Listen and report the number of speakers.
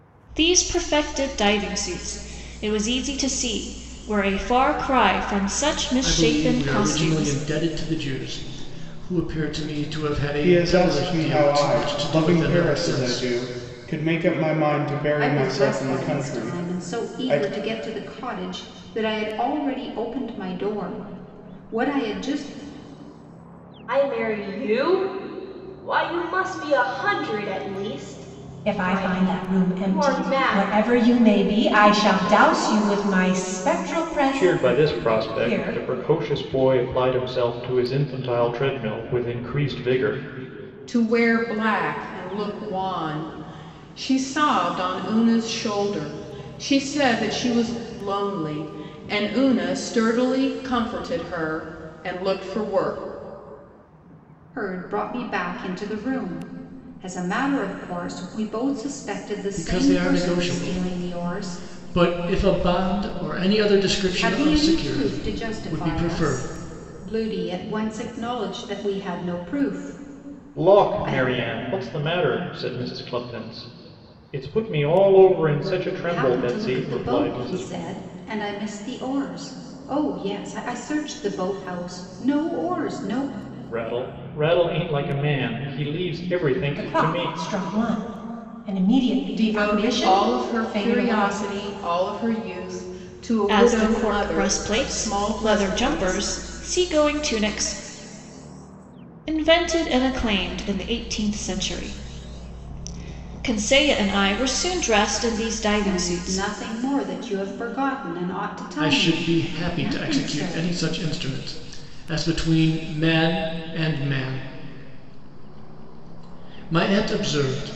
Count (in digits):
8